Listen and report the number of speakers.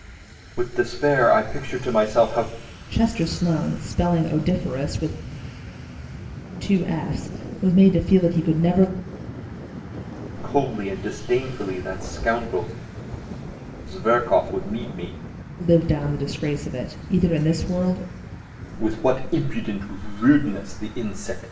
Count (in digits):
2